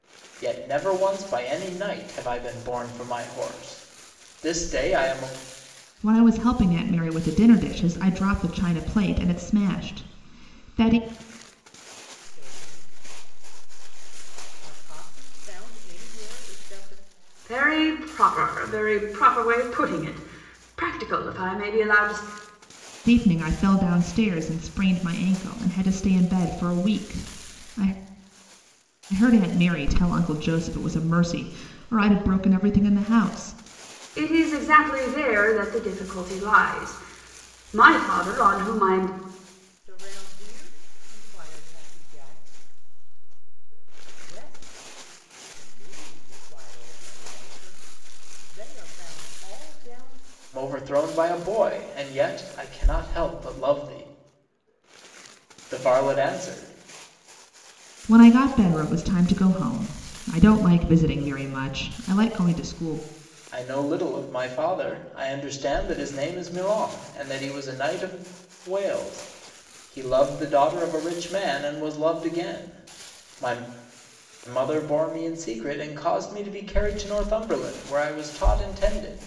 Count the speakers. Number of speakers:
4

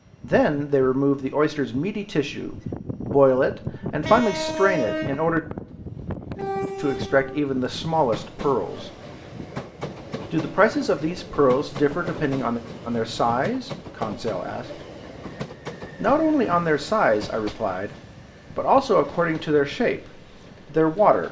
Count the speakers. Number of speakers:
1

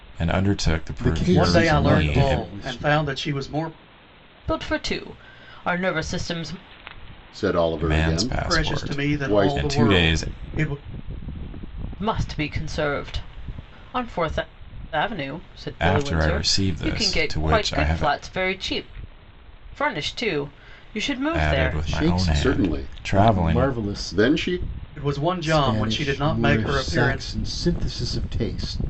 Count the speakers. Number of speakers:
5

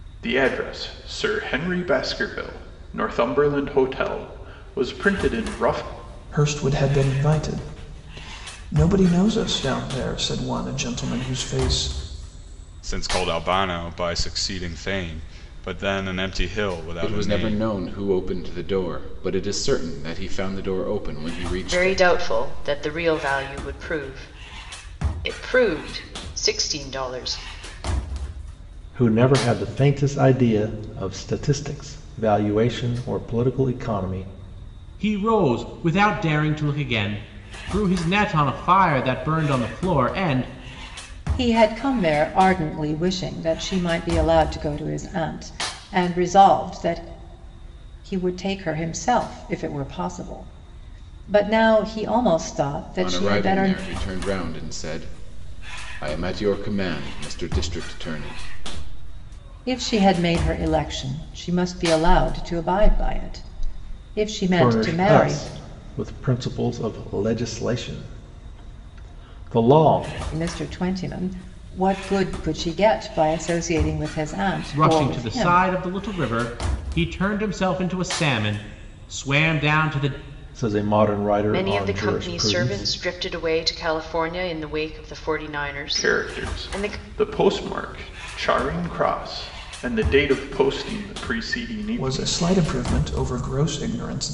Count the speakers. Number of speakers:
8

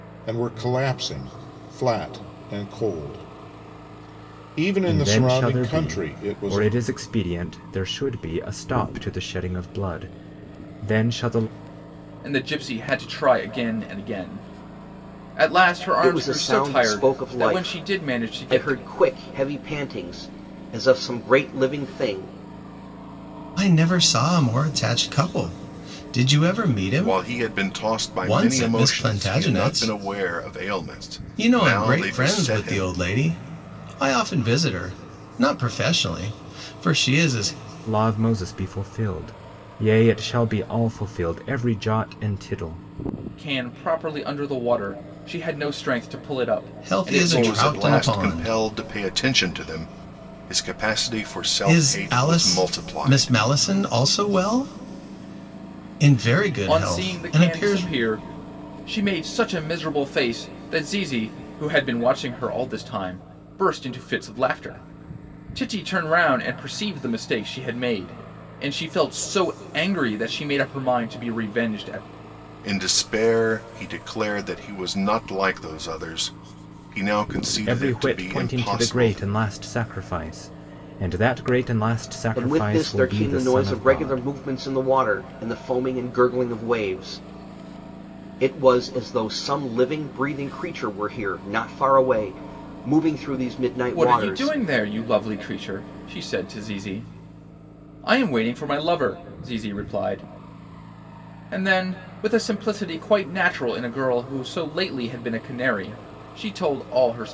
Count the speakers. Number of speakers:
6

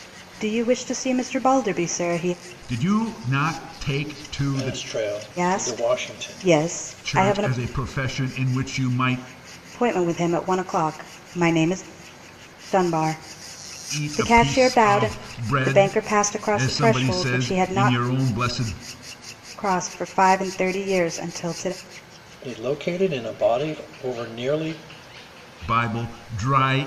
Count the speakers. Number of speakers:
3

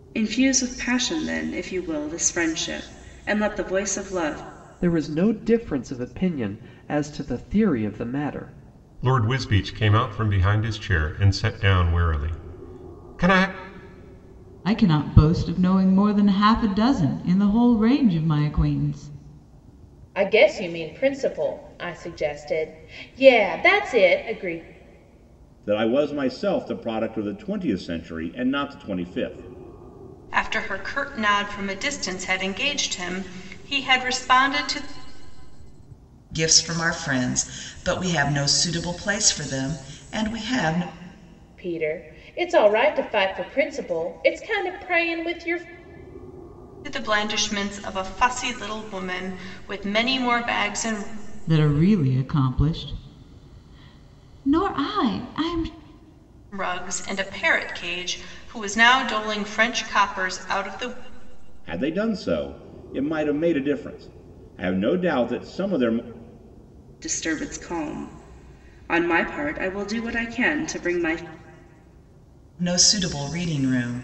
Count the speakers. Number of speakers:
8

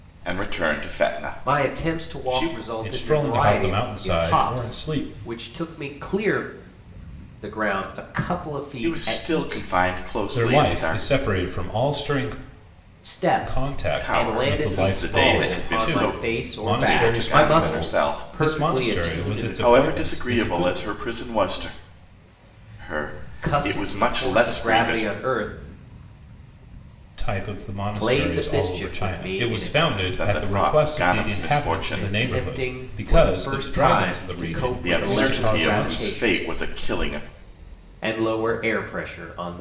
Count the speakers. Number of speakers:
3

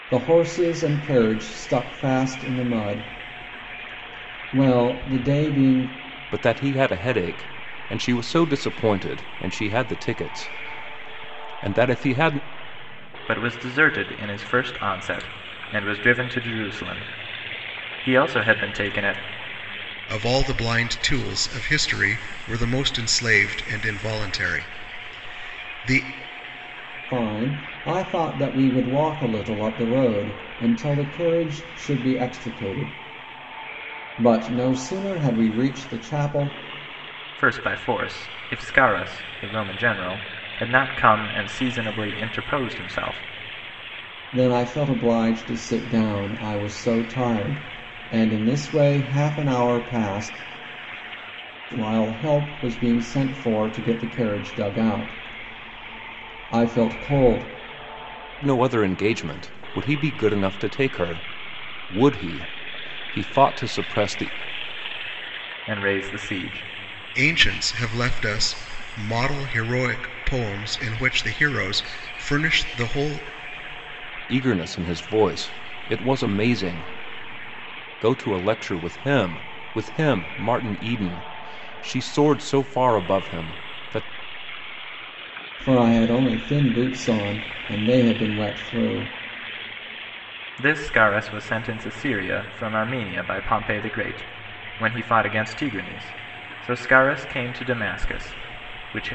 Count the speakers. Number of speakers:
4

